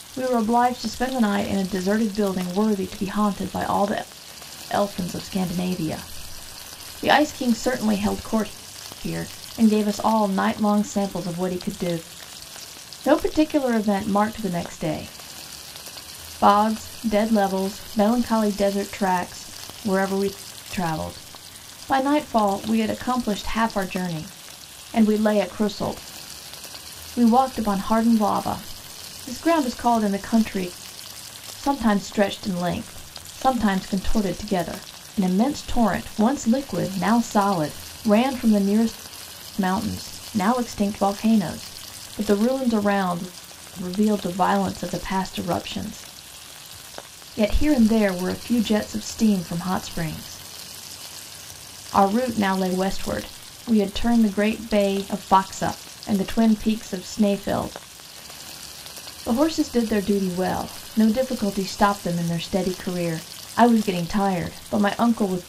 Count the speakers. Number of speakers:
1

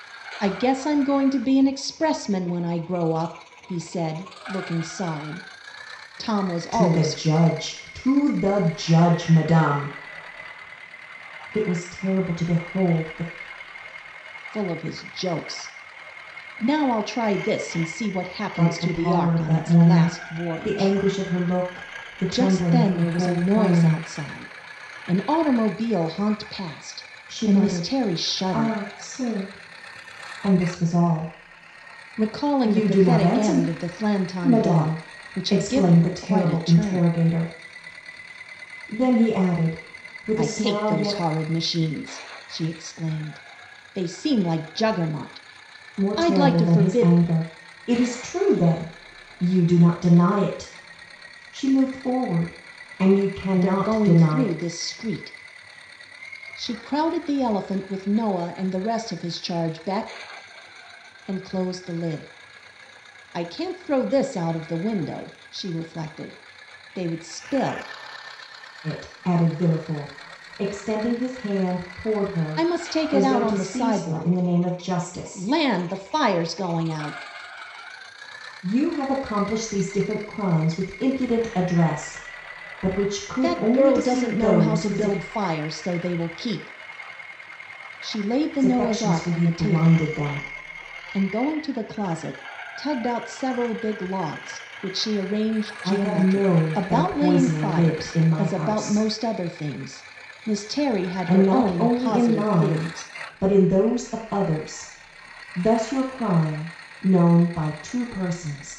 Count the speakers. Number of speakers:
2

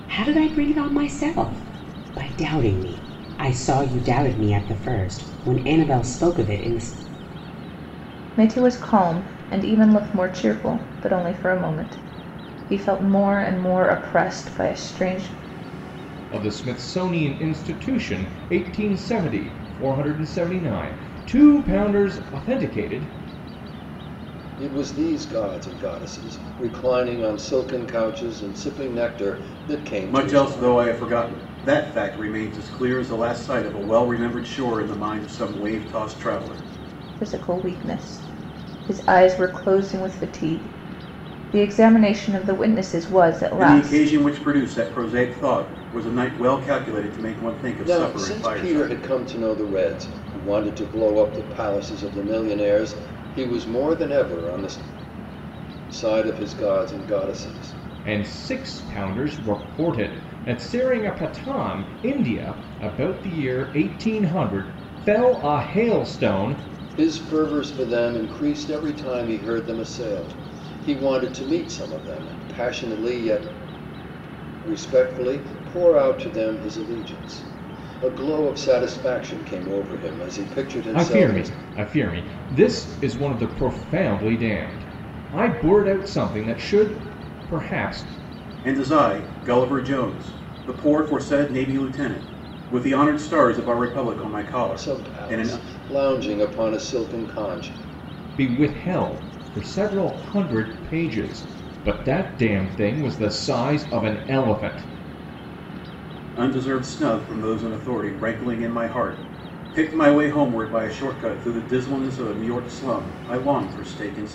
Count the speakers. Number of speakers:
5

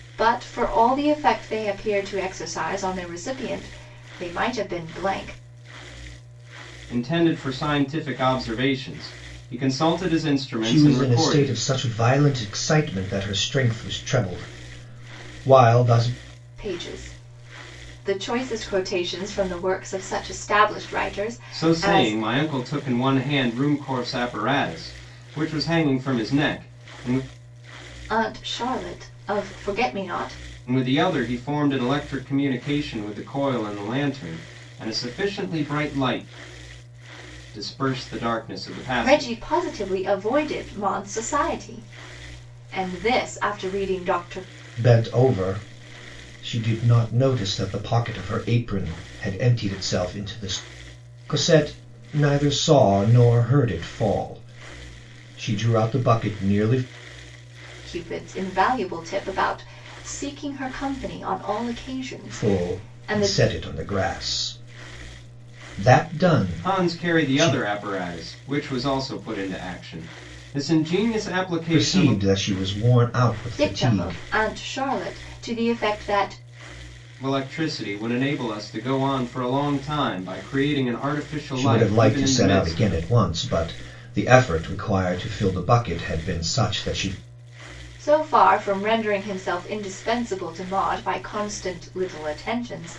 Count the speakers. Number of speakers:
3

